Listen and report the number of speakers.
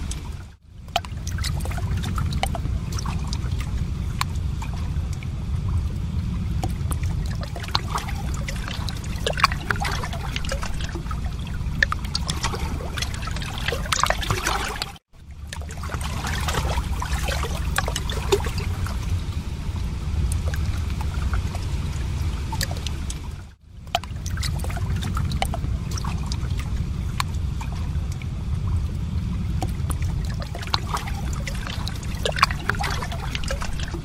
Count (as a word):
zero